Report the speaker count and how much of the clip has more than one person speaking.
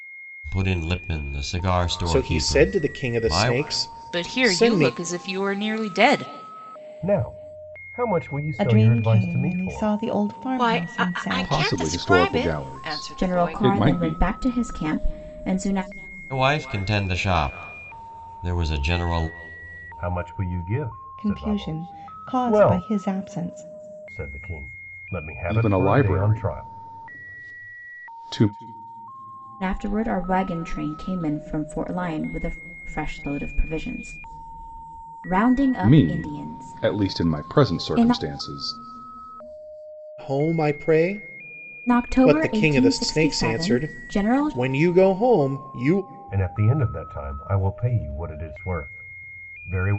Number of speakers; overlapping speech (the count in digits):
8, about 31%